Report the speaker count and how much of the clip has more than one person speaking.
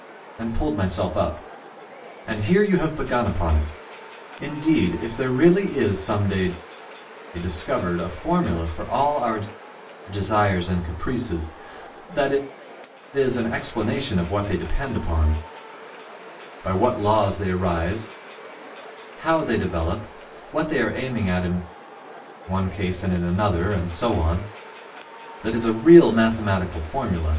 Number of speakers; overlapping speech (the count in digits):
1, no overlap